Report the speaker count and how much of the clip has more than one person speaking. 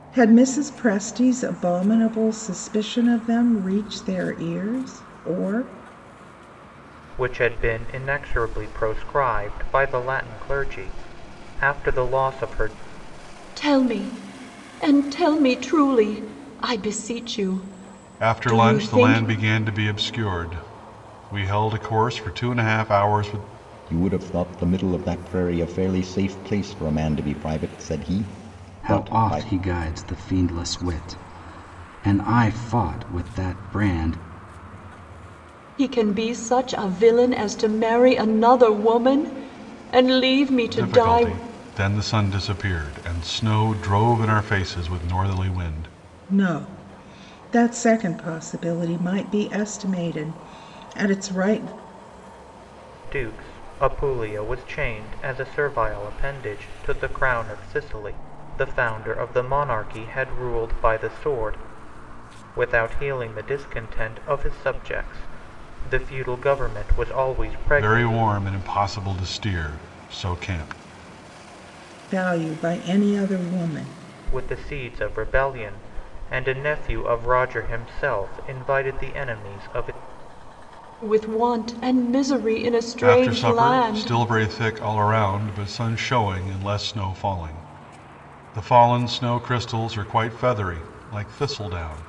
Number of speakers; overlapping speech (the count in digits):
6, about 4%